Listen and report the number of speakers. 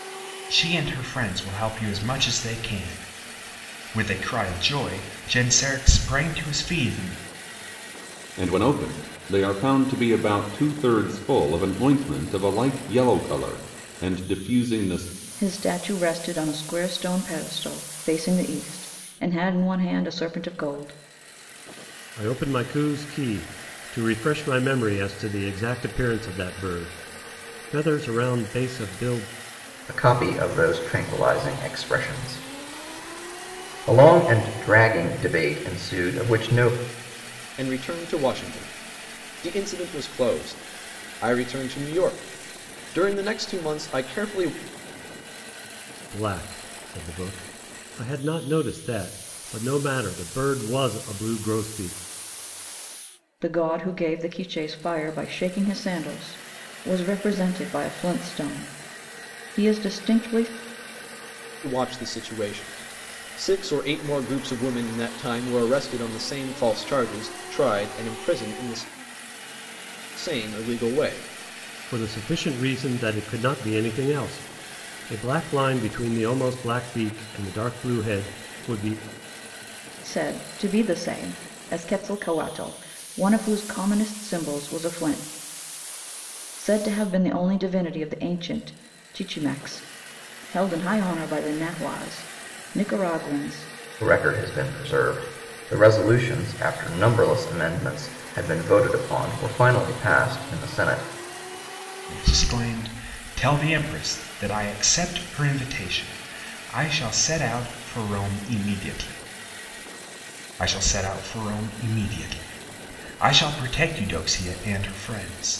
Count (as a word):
six